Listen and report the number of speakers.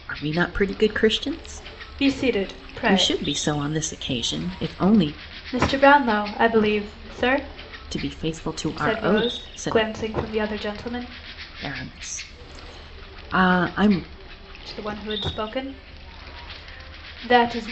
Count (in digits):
2